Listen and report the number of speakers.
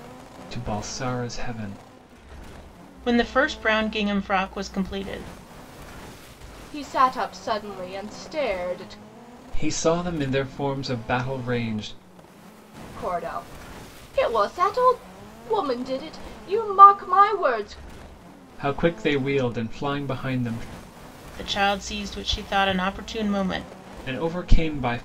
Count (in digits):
3